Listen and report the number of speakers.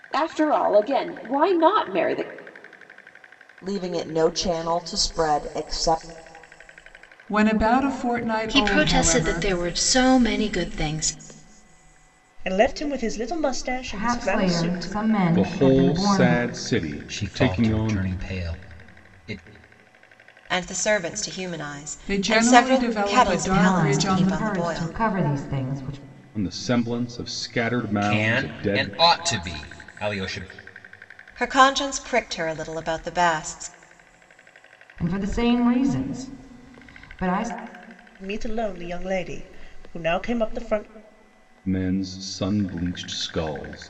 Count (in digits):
9